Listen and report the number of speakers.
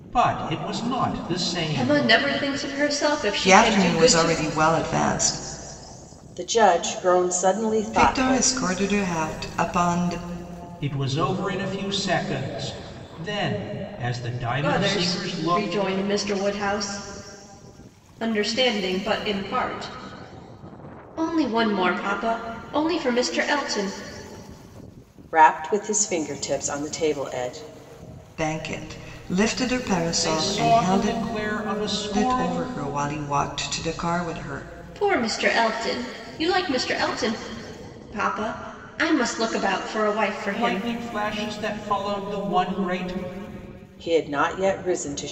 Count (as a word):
four